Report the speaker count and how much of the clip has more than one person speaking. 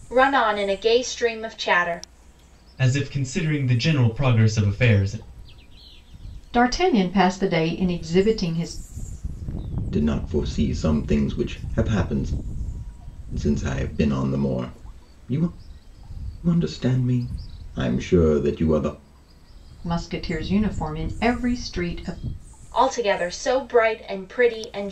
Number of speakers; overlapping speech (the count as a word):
four, no overlap